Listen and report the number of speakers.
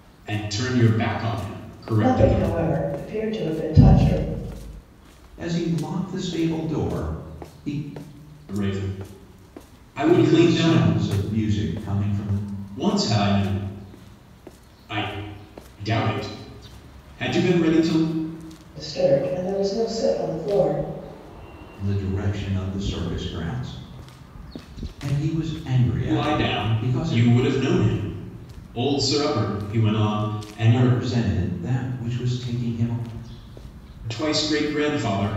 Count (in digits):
3